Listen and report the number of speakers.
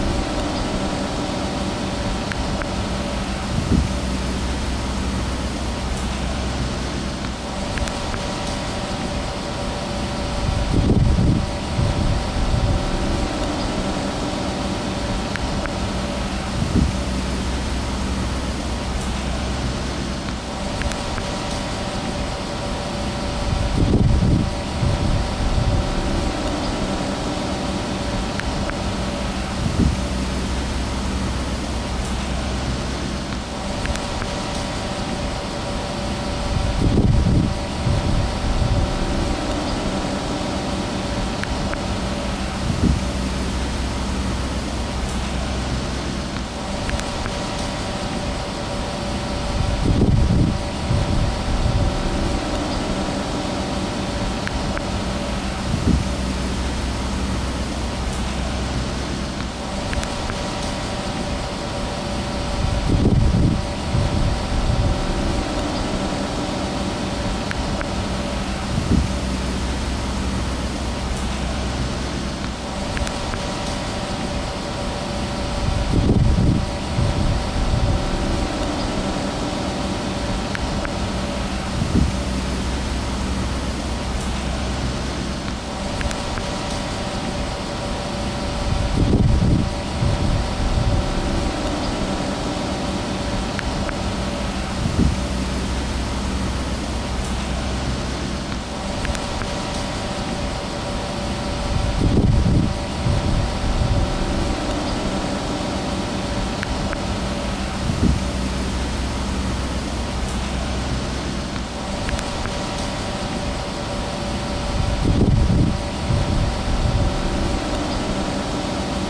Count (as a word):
zero